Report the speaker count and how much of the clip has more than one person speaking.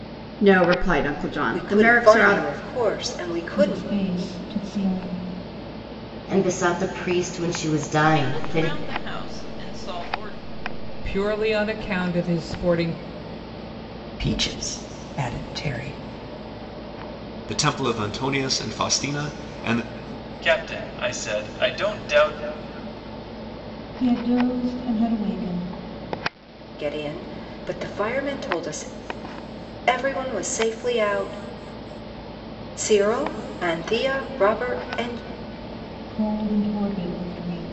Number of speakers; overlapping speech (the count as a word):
nine, about 6%